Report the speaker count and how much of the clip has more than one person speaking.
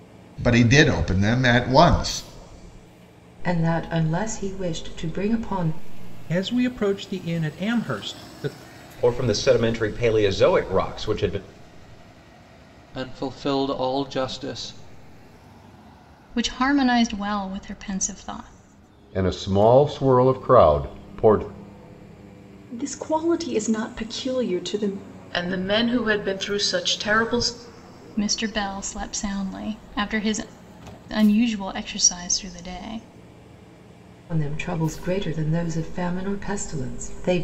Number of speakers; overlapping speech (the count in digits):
9, no overlap